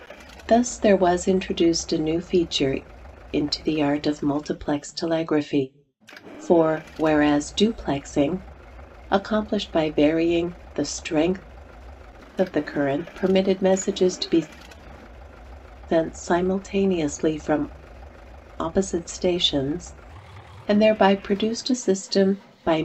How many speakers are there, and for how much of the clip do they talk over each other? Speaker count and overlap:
1, no overlap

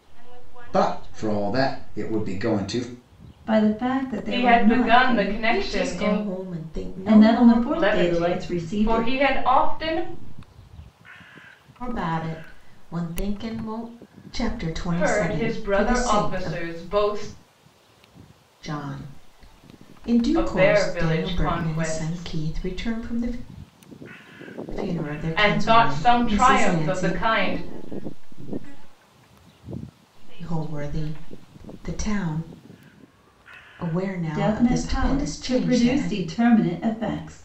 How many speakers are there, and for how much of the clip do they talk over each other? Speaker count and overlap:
5, about 42%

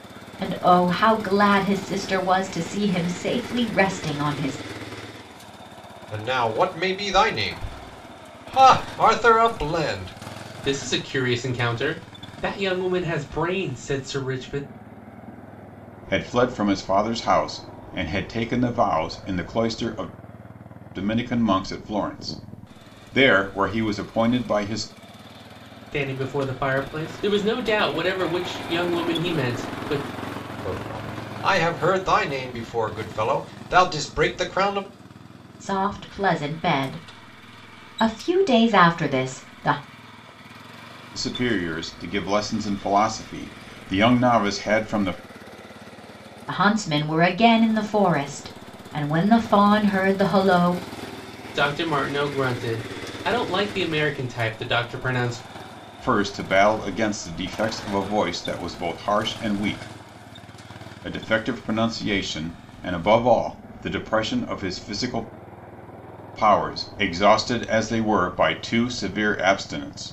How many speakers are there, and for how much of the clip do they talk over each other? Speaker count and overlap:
4, no overlap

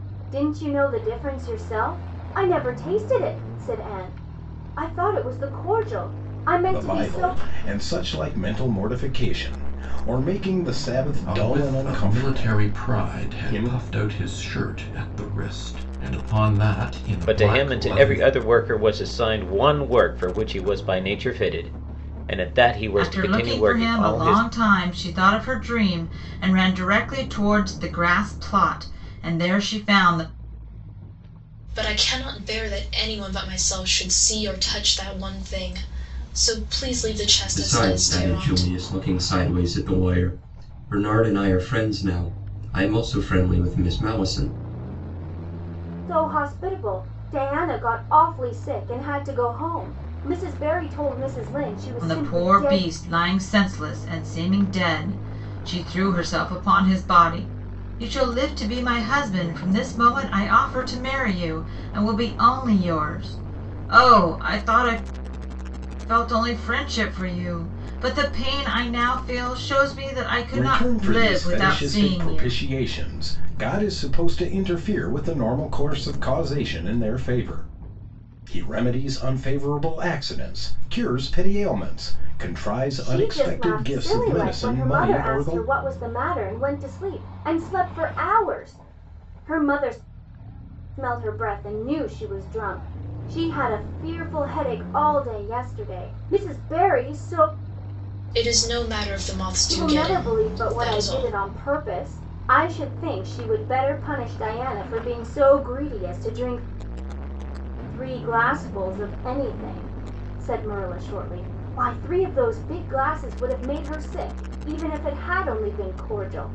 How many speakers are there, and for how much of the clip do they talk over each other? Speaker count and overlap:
7, about 12%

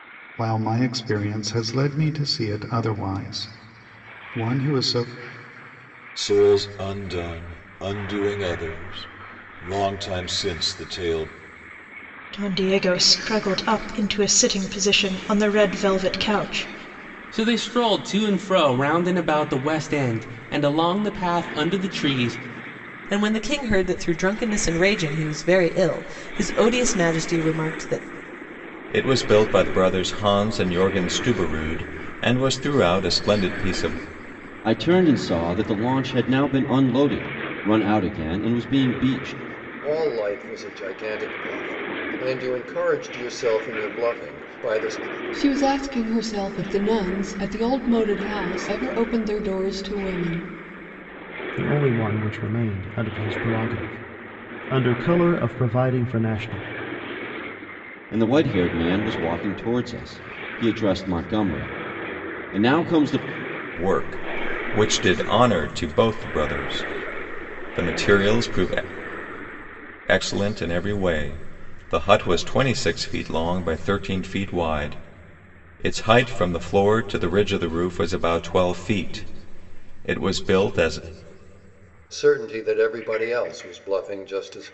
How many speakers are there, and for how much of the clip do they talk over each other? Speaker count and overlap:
10, no overlap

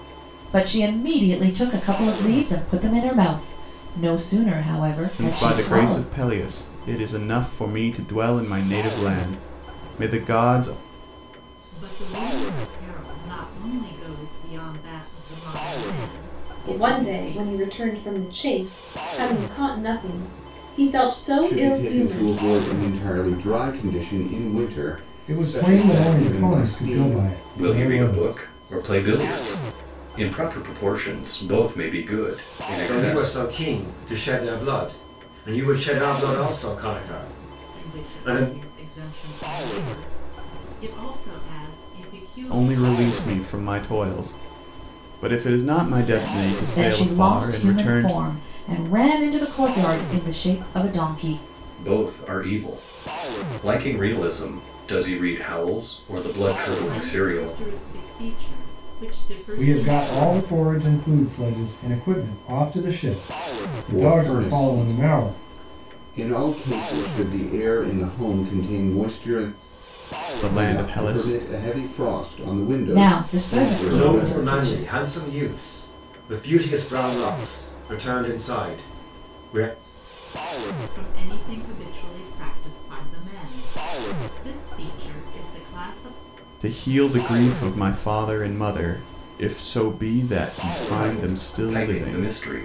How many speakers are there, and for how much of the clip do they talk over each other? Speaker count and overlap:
8, about 19%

